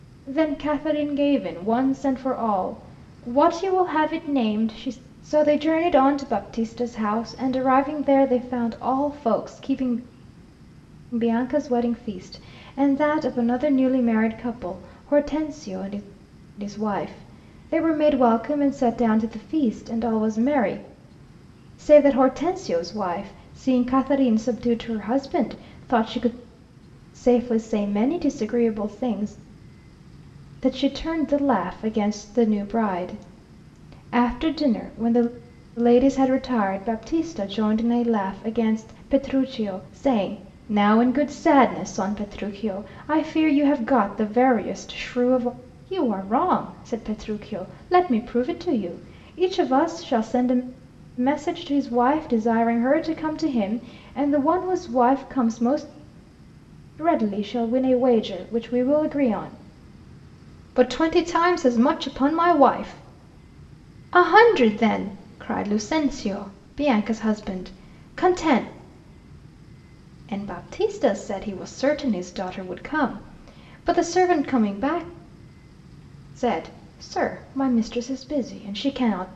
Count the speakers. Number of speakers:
one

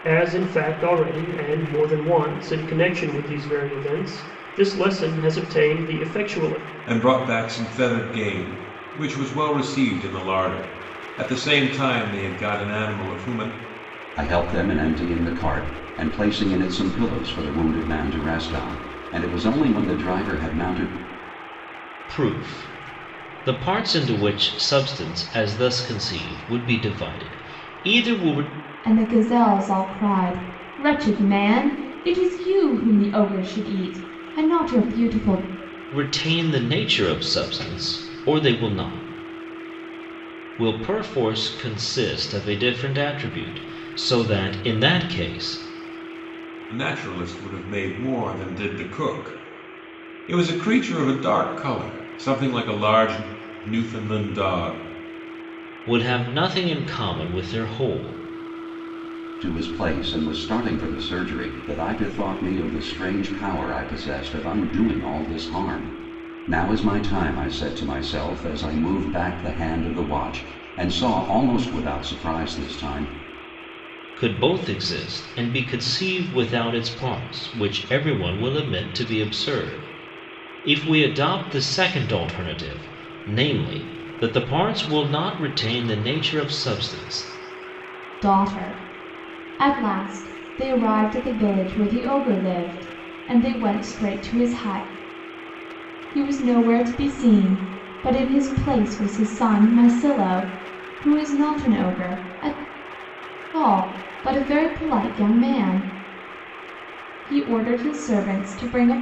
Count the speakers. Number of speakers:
five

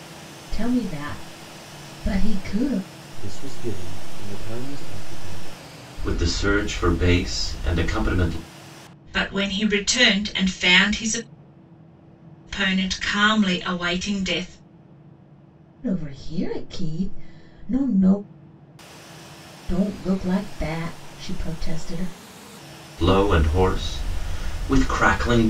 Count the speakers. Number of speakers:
four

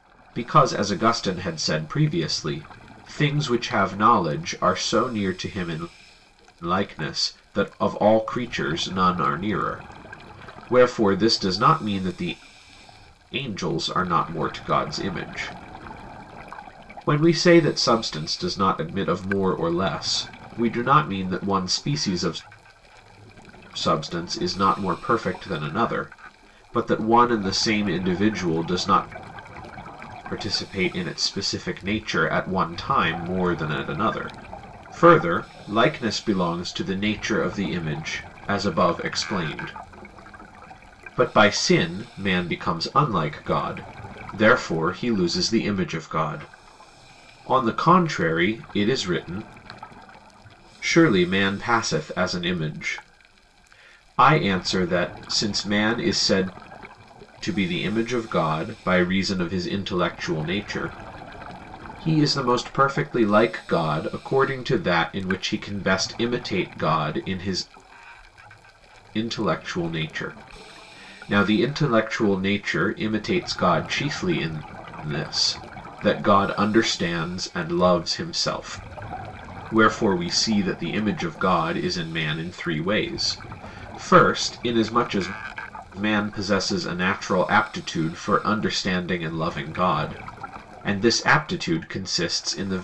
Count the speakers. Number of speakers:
one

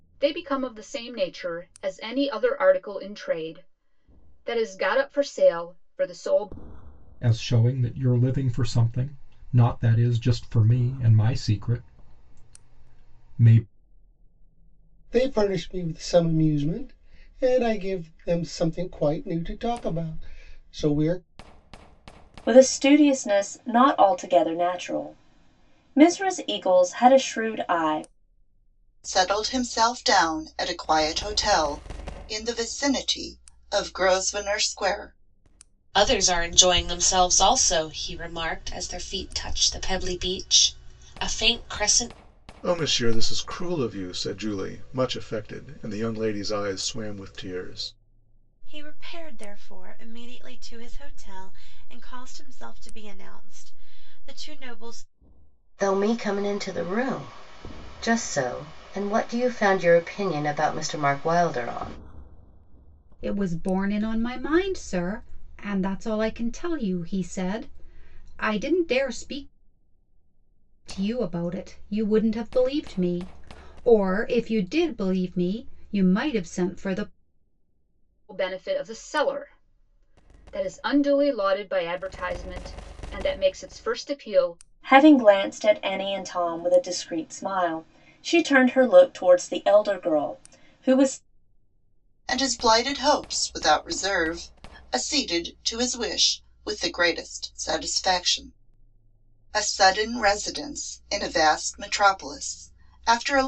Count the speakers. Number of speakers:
ten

